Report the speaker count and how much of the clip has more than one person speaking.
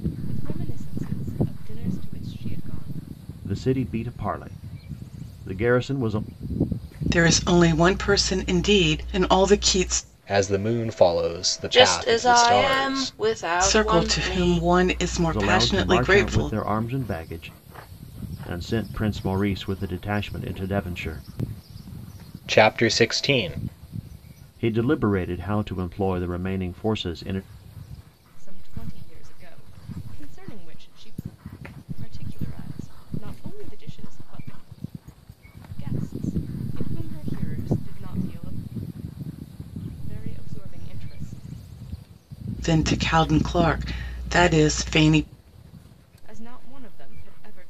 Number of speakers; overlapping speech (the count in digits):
5, about 8%